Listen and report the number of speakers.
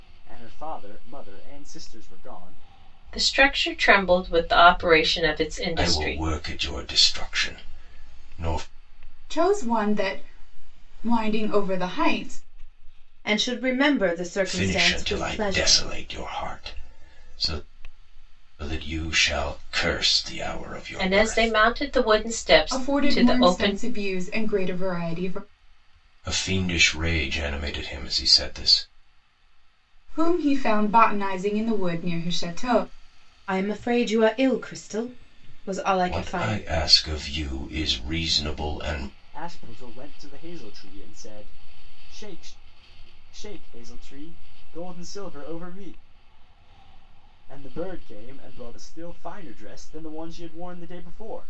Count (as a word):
five